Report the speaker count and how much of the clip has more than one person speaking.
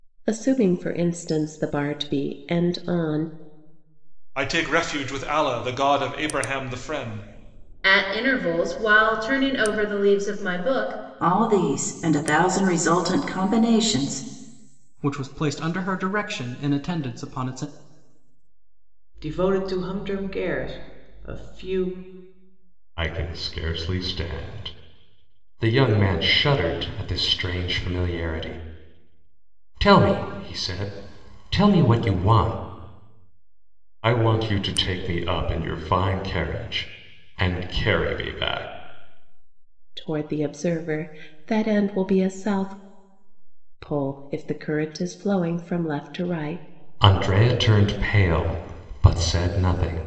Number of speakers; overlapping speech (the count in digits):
7, no overlap